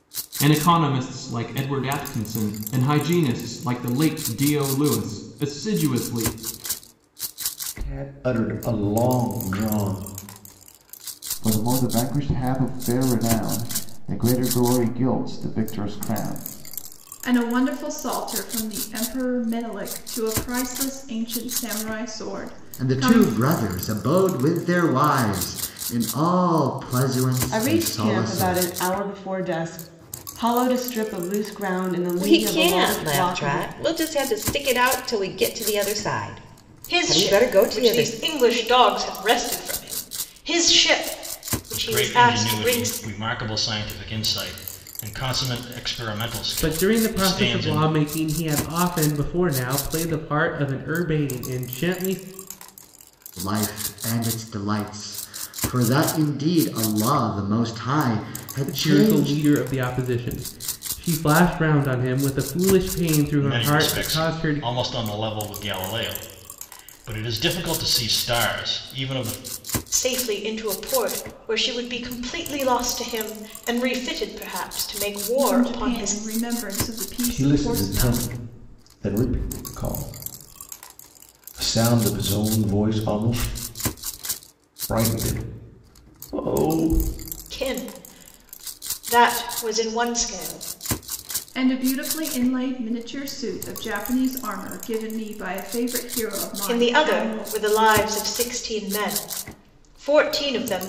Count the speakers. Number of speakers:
ten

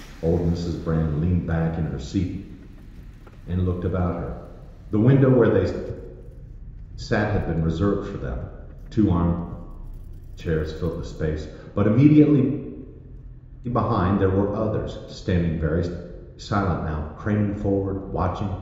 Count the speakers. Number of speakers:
one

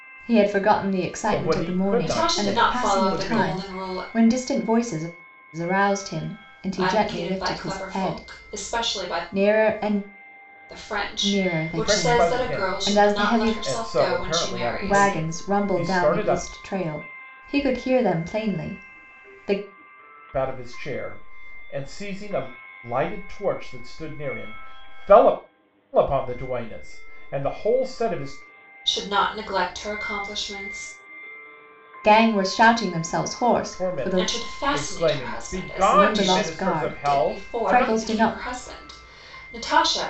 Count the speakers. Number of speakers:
three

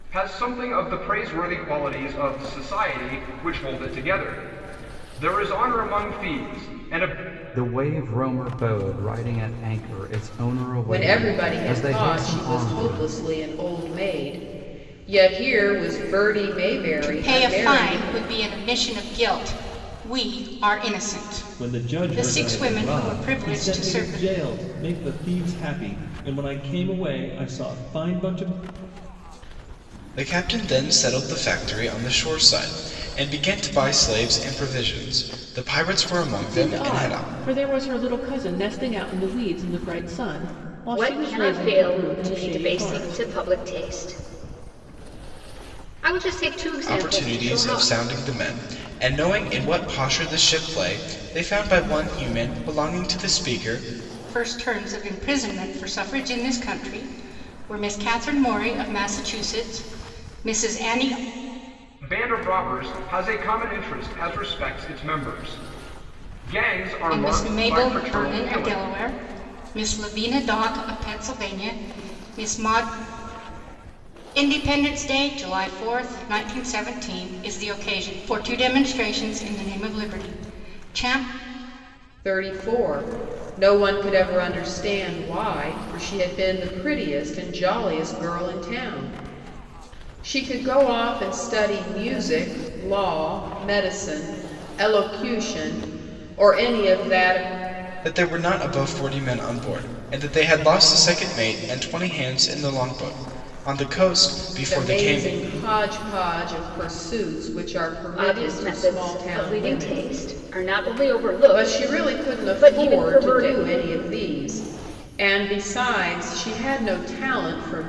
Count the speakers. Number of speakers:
eight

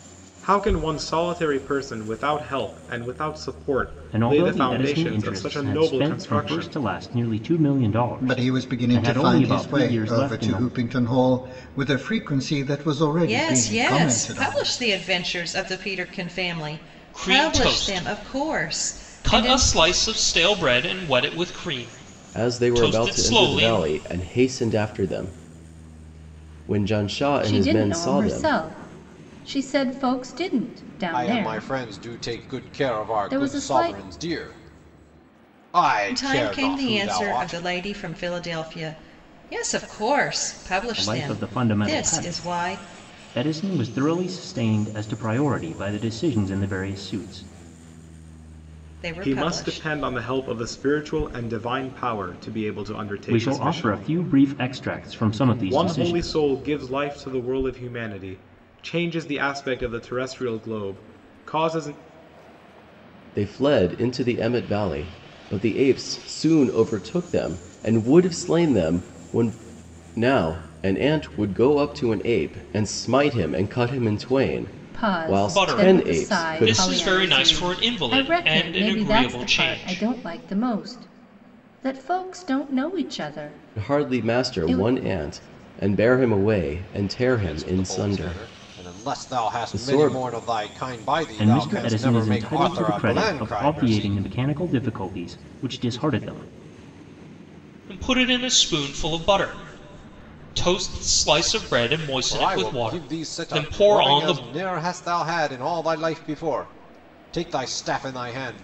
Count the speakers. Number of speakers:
eight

